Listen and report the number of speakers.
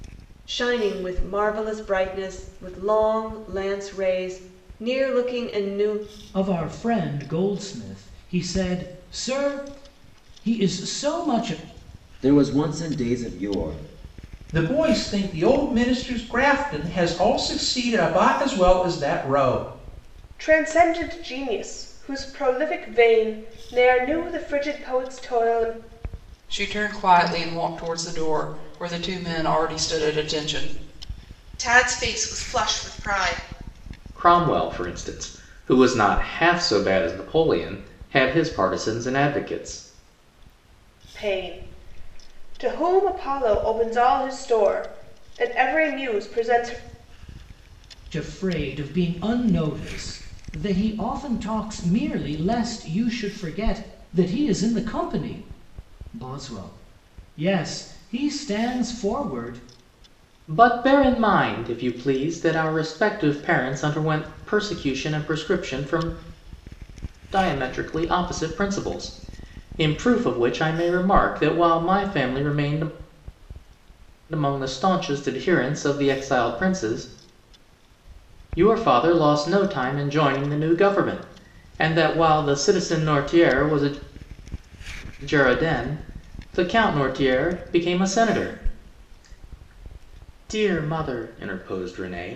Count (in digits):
8